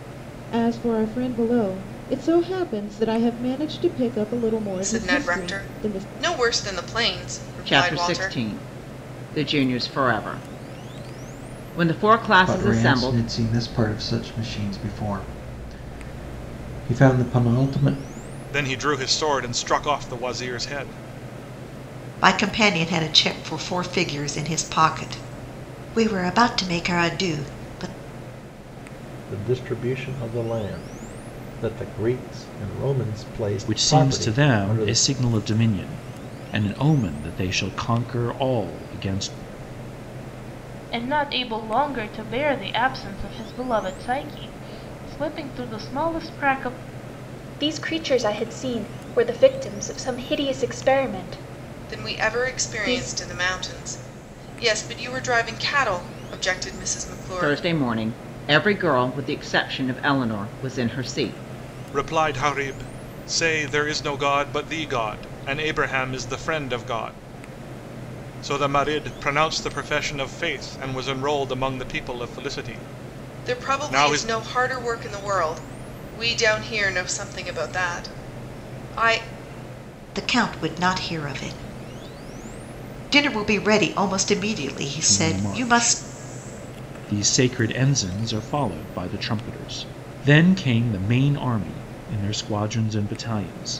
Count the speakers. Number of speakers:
10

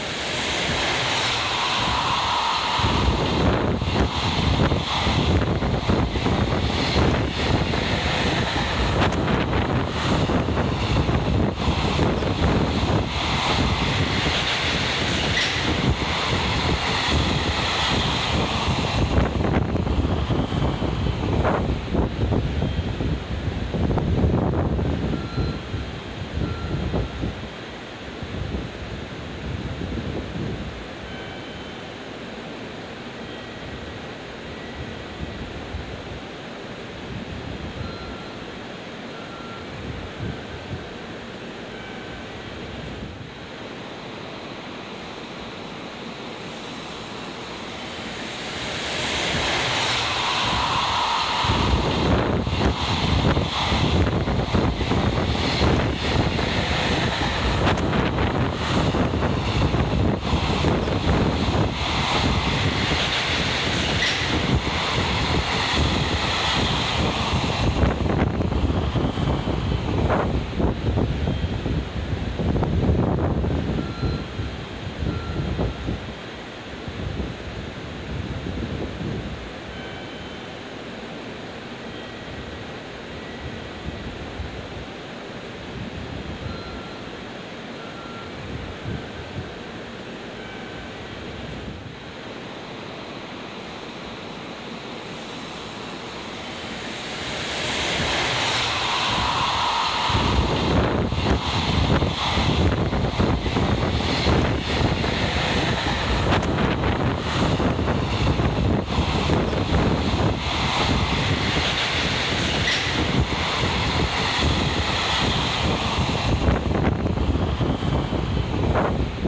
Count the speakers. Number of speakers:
0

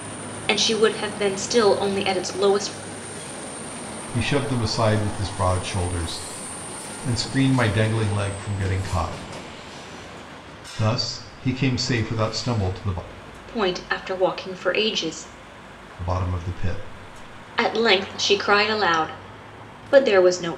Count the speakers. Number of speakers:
2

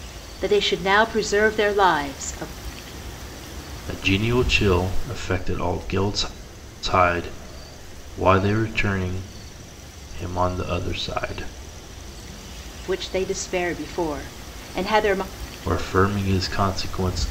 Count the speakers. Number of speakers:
2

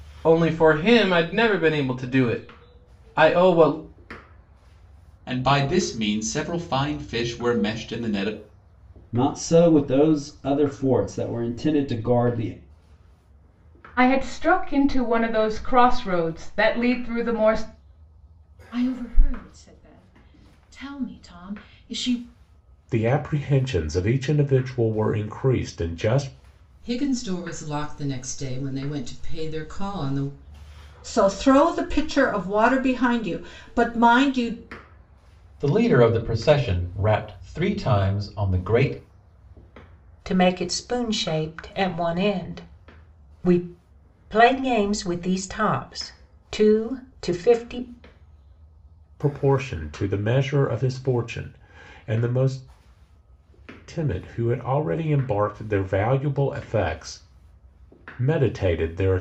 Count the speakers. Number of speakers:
10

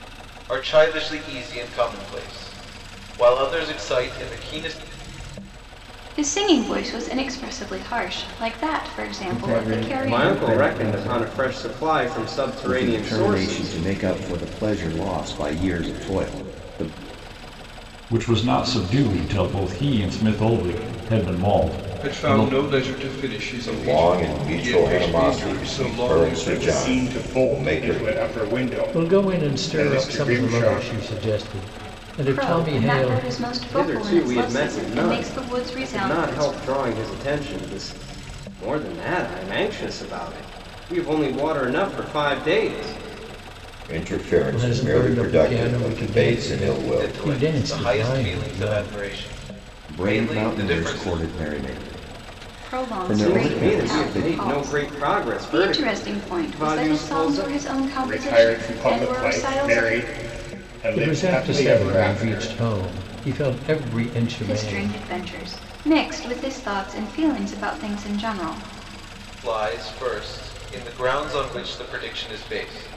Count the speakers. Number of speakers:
10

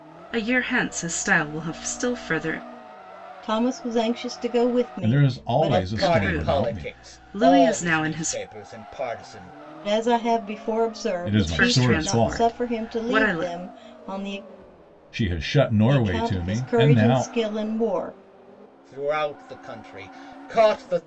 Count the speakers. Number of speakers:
4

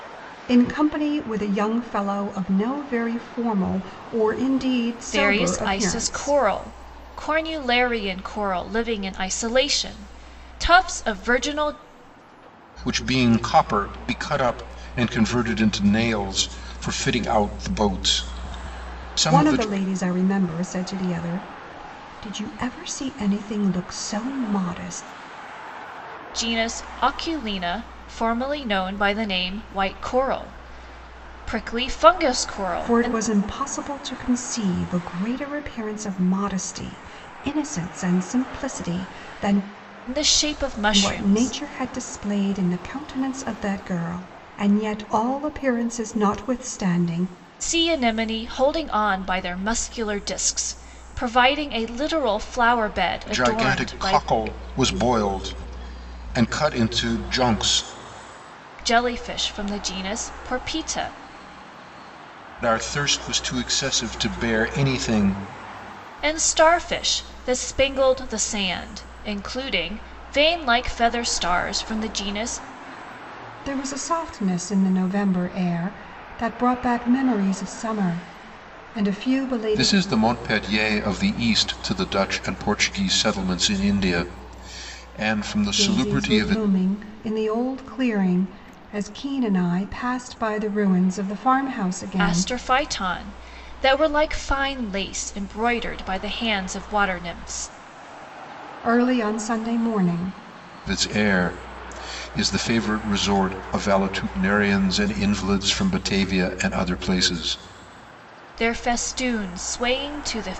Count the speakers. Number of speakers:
3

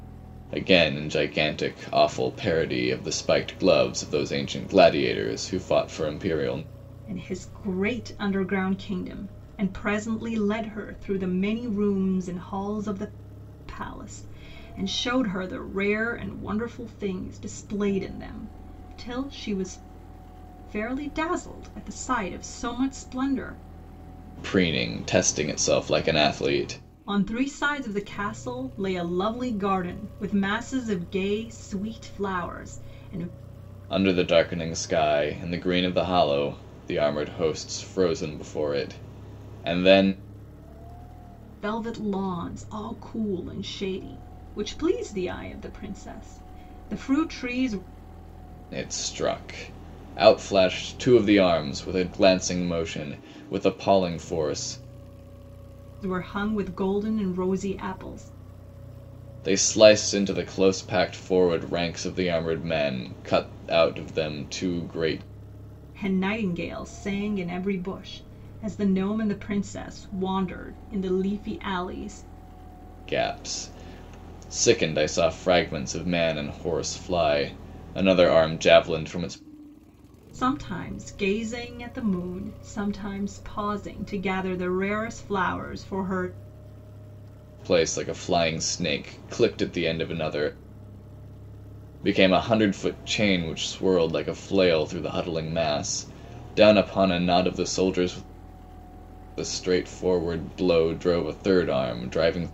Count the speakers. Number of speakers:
2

